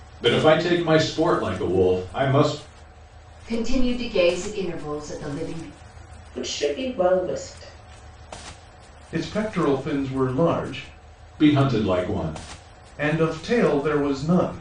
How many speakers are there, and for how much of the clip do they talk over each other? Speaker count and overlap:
4, no overlap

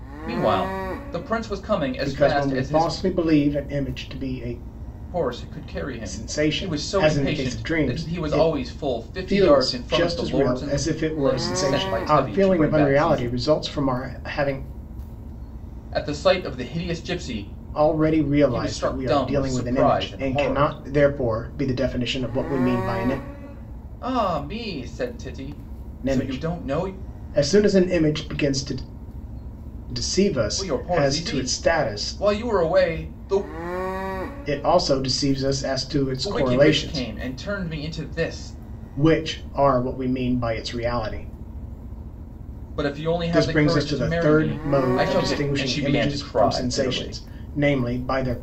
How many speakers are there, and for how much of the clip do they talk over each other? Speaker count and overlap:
2, about 34%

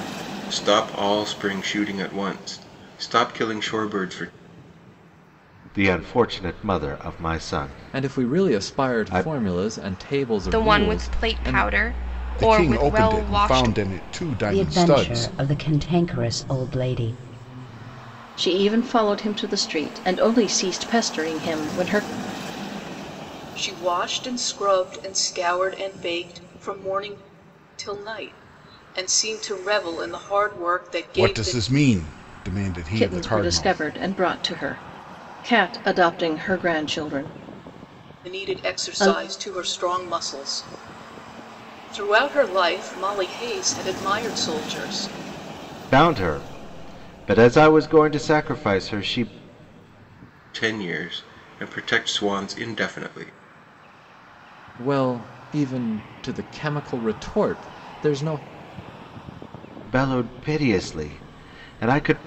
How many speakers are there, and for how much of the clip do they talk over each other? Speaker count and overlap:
8, about 12%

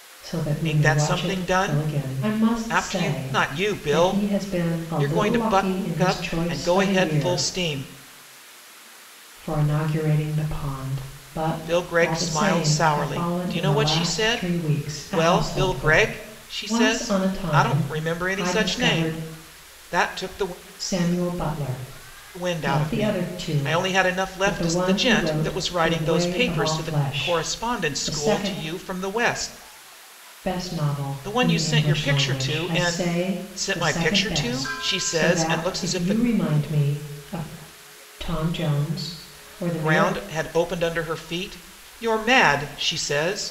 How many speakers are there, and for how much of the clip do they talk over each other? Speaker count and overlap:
2, about 56%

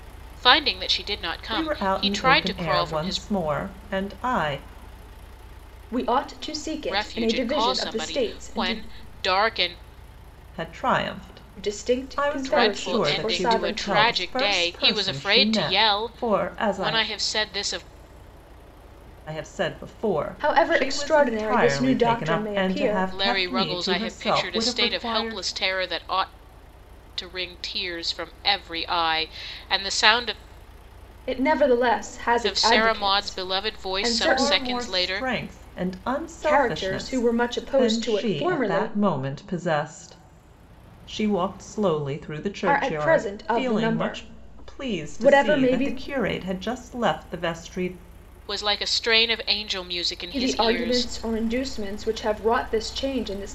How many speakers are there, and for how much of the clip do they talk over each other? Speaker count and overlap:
3, about 43%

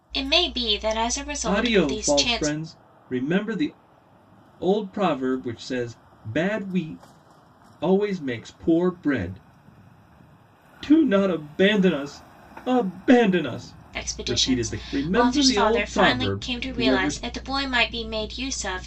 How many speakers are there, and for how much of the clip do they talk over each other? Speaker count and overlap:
2, about 23%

